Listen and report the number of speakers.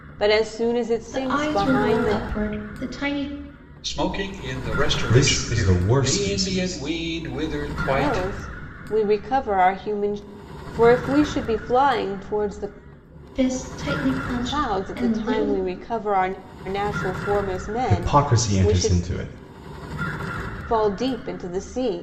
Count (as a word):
four